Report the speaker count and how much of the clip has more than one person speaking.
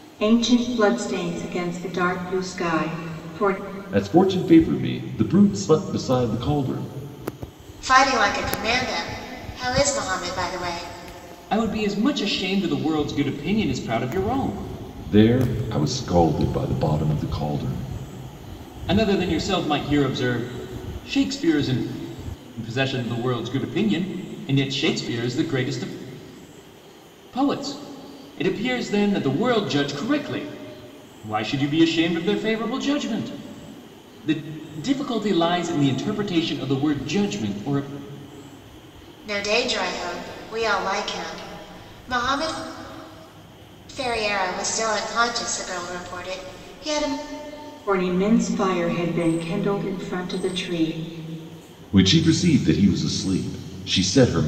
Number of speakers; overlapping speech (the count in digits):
4, no overlap